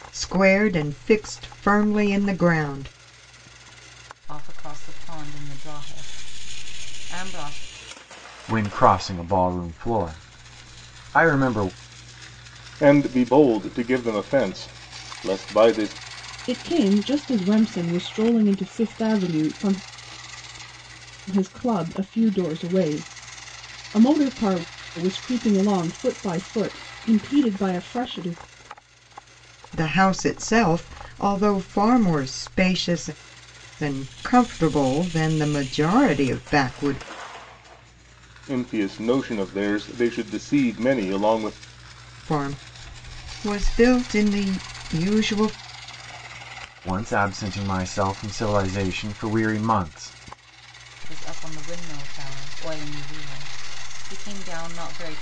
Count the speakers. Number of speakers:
5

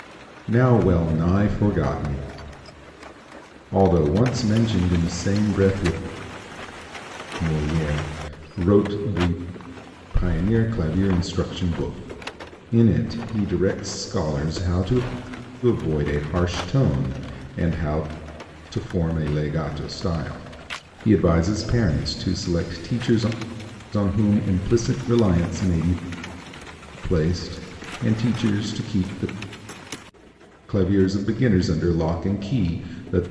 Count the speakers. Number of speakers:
1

